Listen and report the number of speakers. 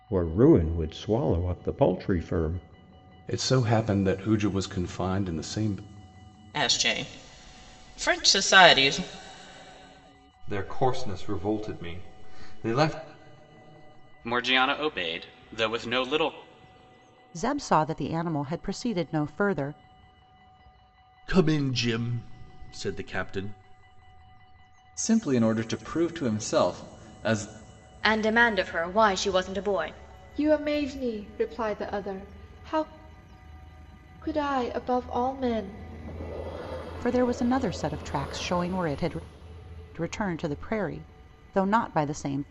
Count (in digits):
10